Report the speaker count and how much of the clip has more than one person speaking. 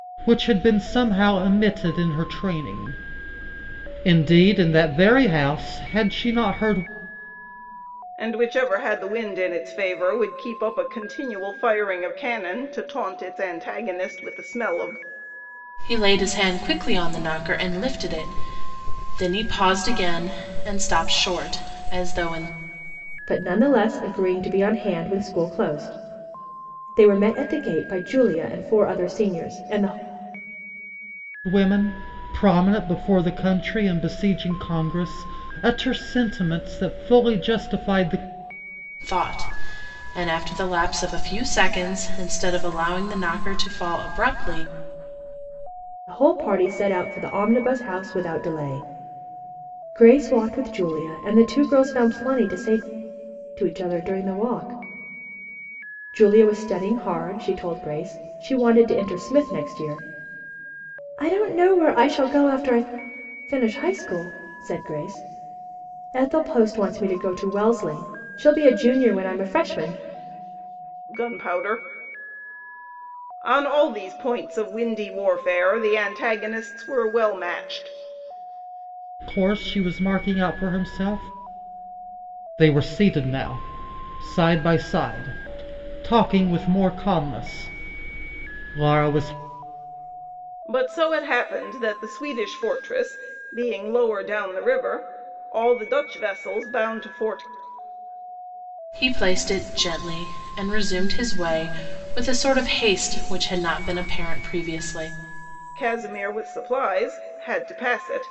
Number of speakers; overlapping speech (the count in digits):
4, no overlap